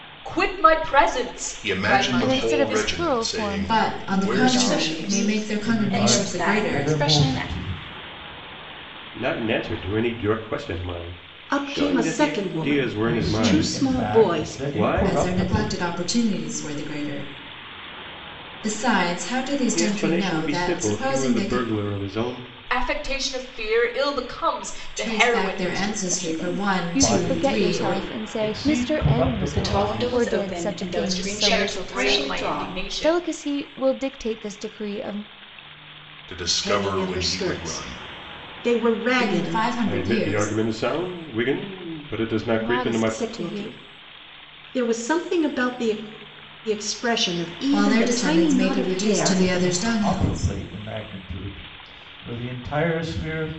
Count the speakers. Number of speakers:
8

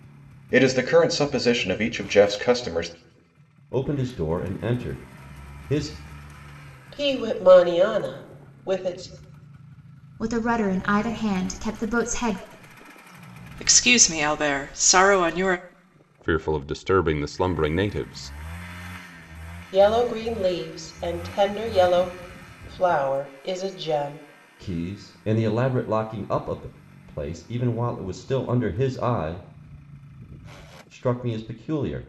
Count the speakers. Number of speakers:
6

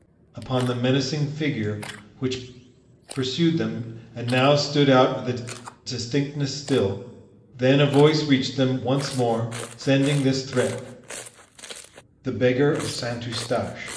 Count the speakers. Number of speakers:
1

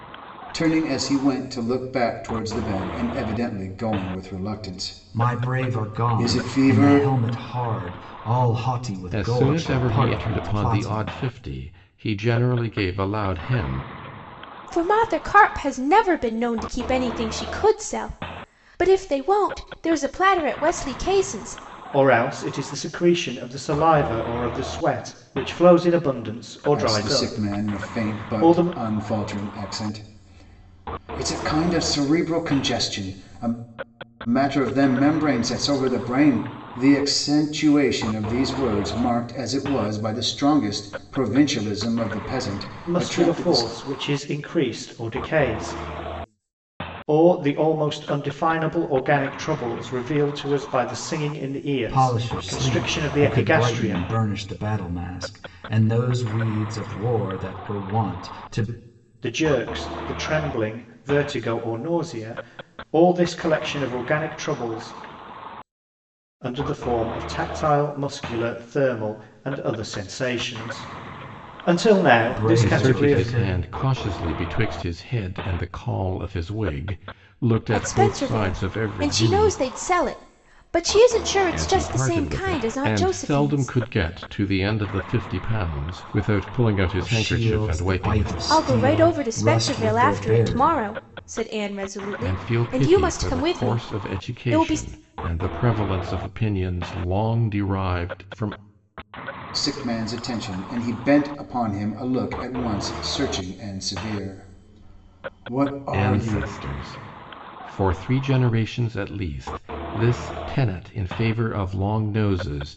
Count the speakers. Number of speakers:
5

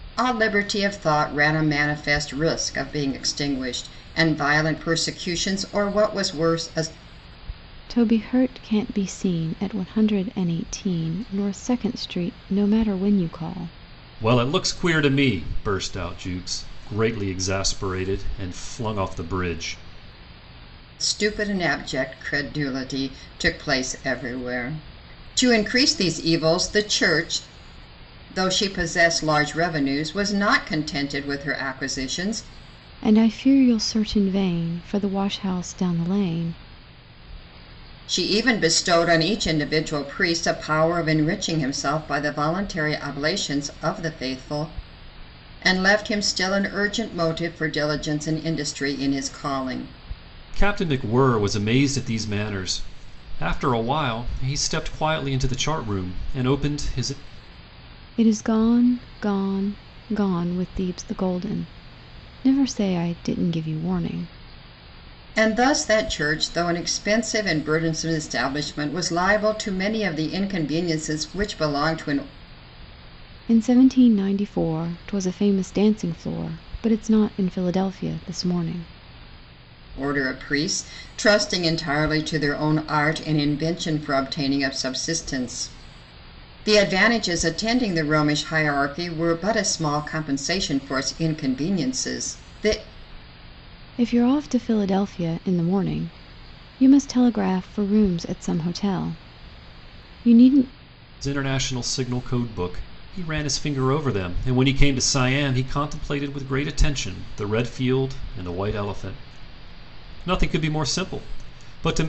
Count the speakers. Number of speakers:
3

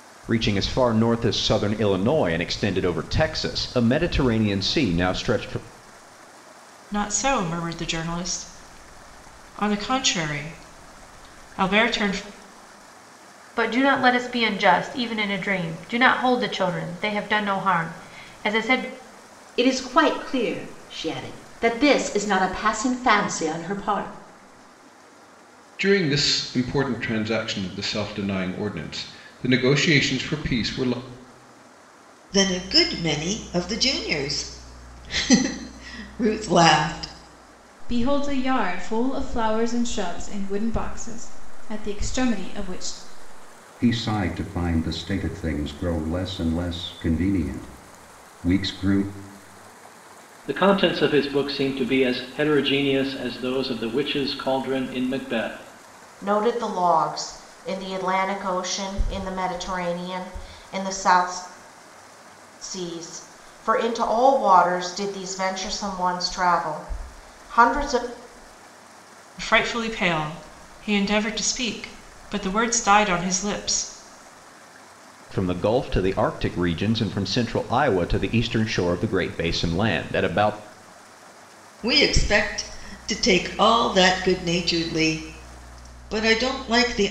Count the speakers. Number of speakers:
10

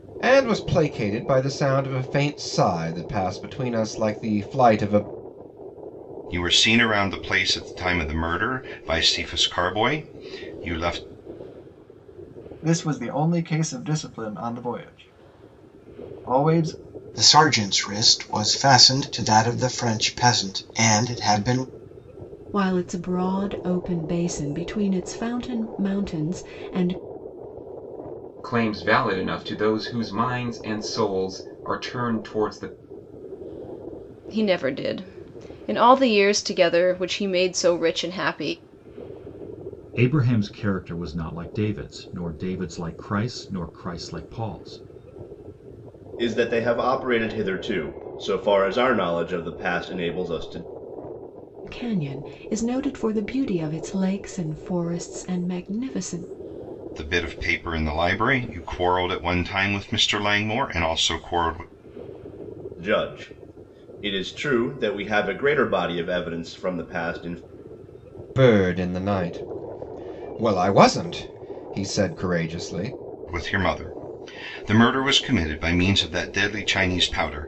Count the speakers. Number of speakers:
9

